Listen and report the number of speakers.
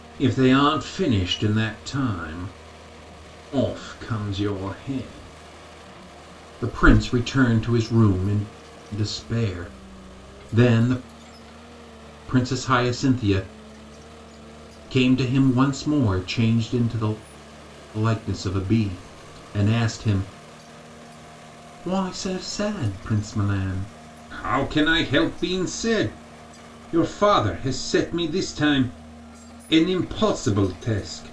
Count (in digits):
1